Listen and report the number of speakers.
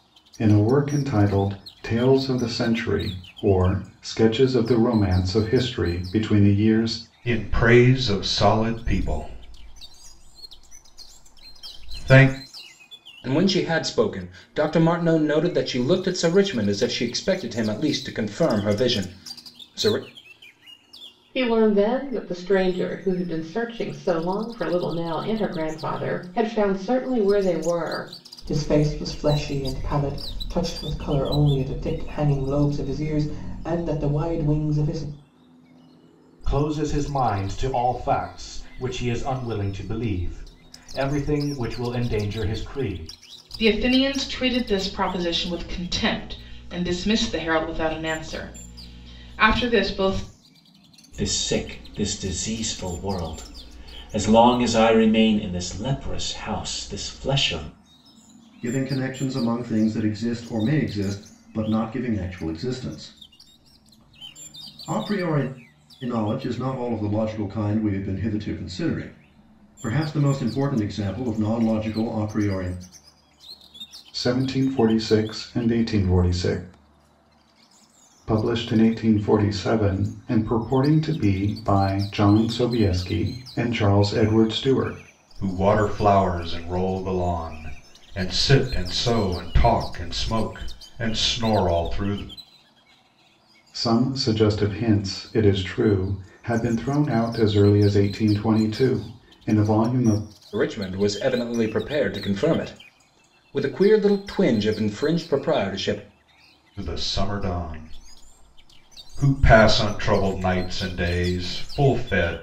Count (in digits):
9